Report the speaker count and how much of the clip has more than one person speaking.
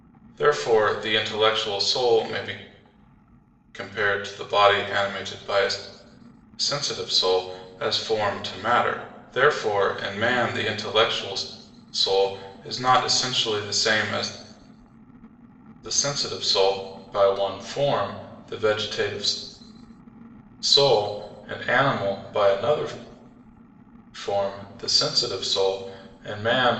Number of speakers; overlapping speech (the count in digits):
1, no overlap